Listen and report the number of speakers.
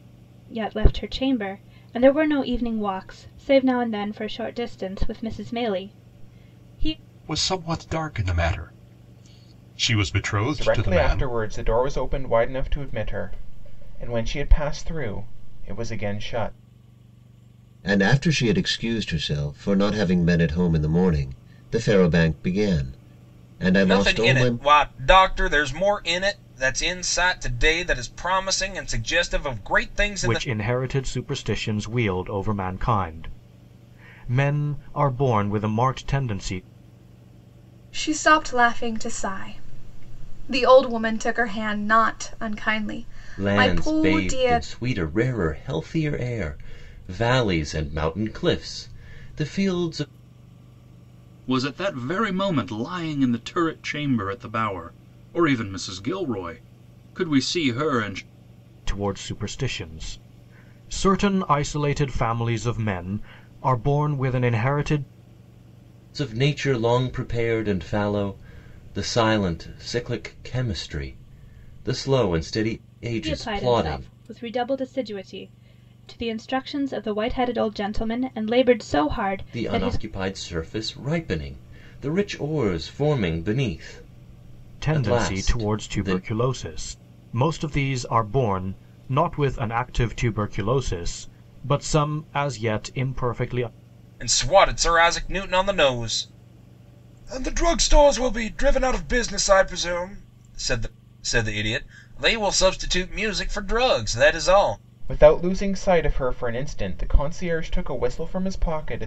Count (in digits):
9